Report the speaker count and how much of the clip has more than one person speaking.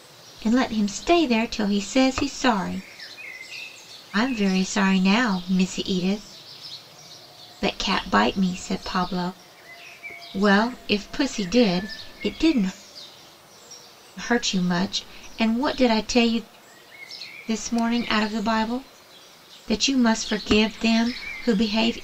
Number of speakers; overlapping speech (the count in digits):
1, no overlap